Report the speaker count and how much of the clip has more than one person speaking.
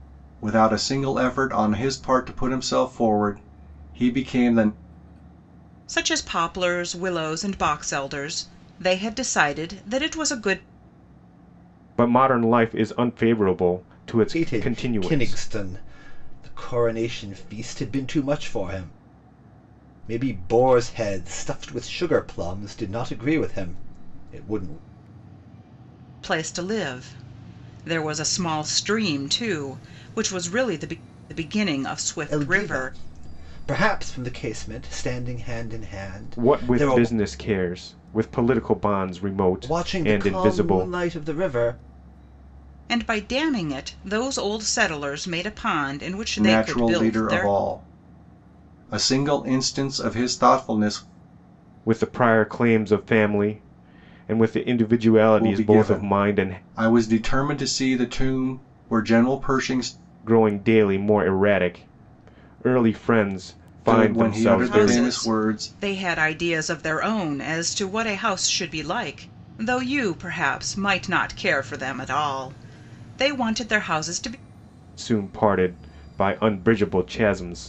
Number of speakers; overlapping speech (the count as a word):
four, about 11%